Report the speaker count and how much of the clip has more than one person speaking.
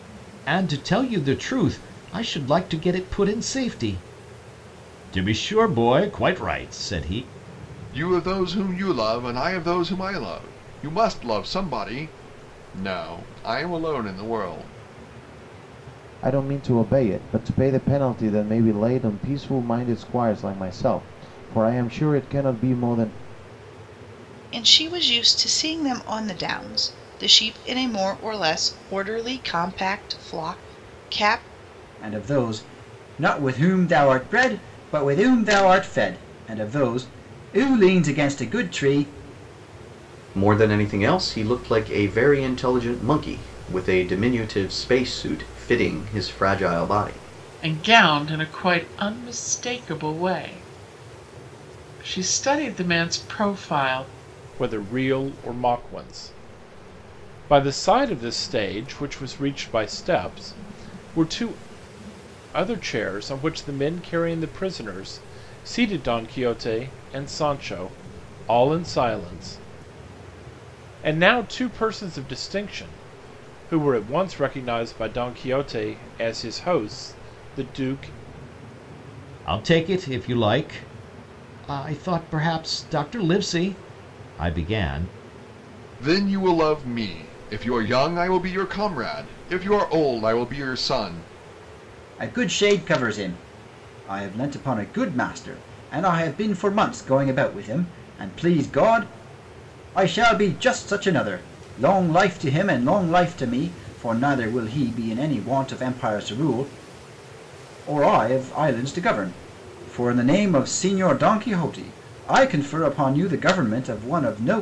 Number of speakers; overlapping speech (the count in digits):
8, no overlap